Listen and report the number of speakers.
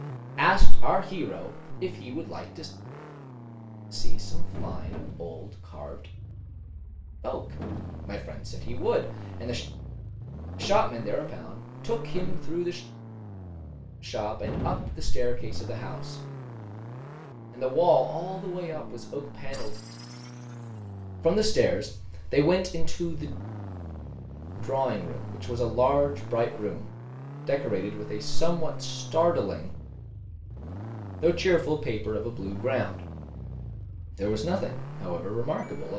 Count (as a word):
one